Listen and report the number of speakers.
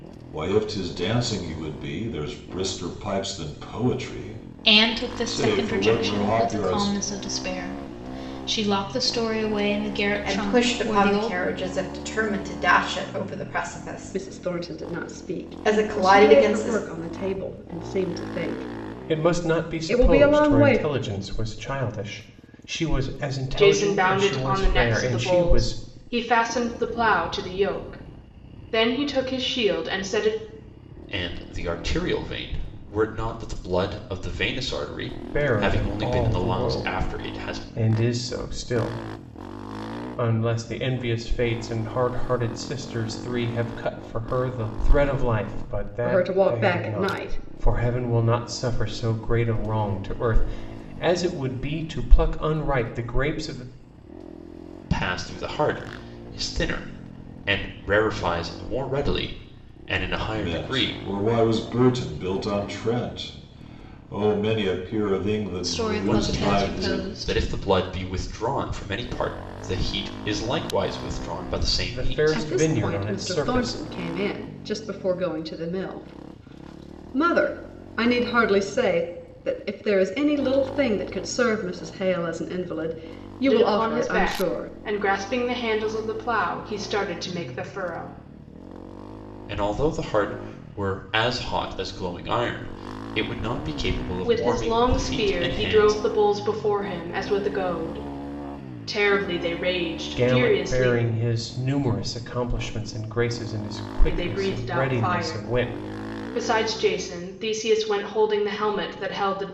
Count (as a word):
seven